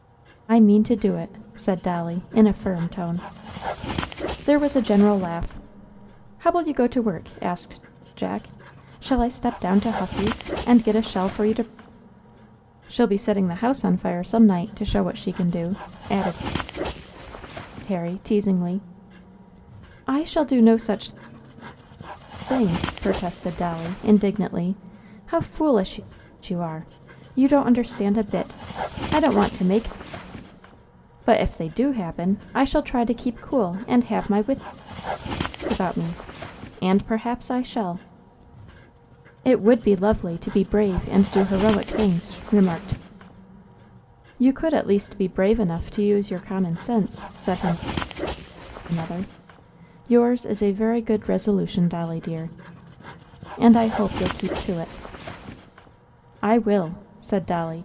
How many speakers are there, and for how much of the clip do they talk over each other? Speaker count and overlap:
1, no overlap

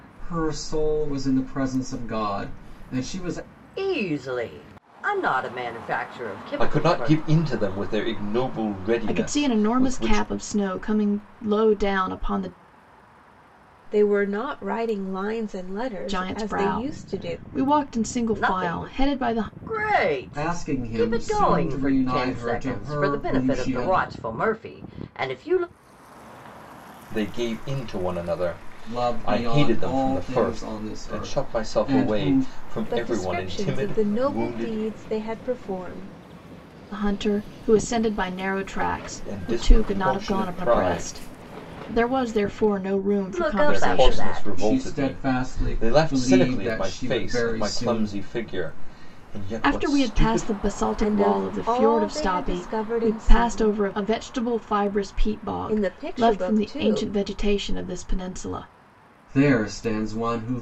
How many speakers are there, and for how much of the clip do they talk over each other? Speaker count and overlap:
5, about 41%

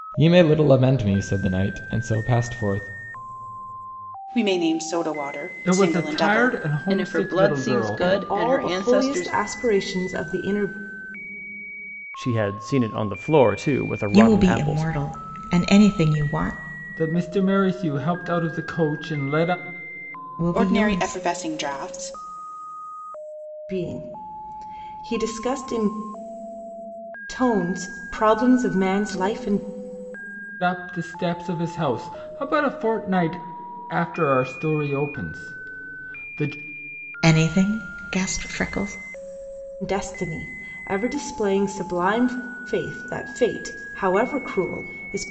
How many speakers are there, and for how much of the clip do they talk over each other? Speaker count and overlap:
7, about 11%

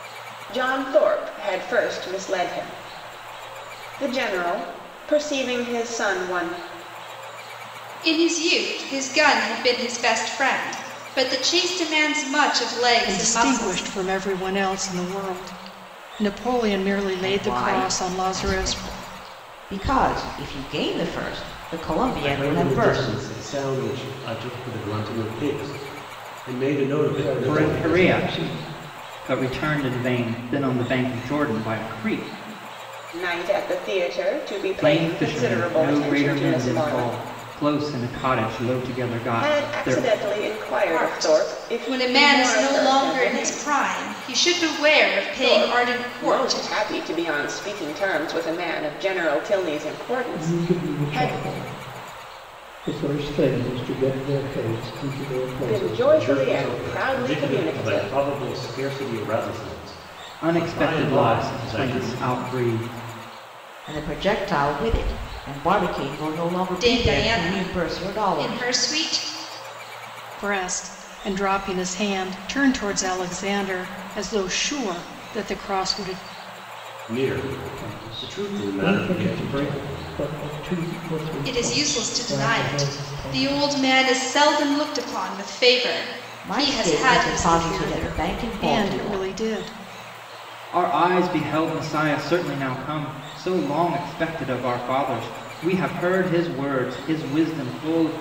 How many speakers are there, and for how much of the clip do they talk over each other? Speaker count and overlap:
7, about 28%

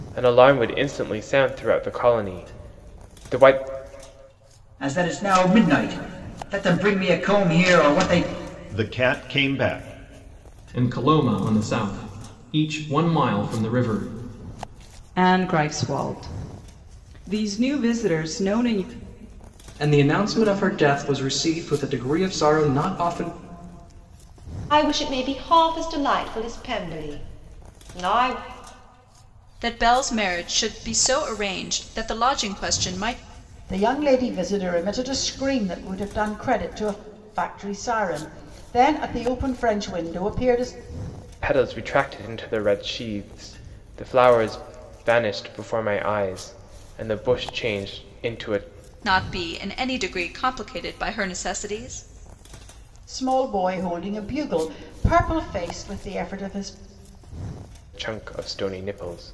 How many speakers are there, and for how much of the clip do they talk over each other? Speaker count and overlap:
9, no overlap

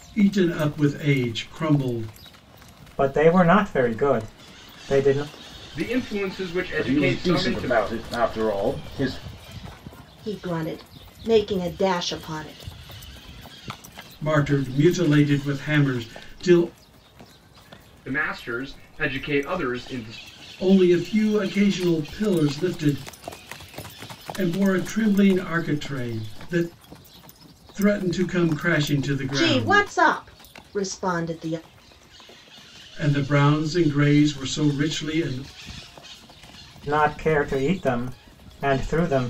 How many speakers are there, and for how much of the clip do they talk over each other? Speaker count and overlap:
5, about 4%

